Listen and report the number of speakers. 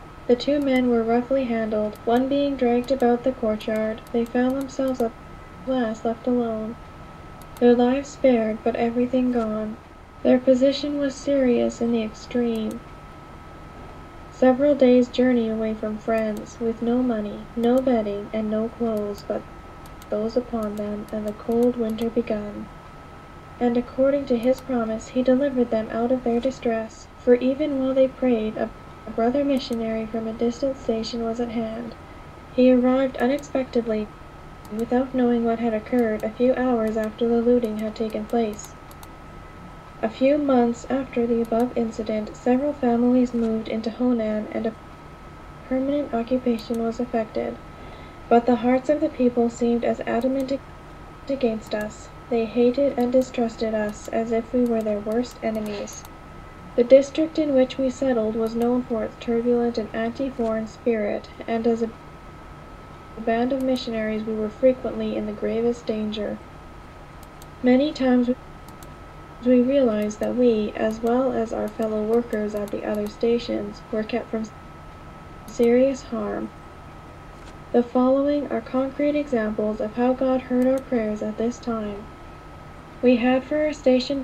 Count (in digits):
1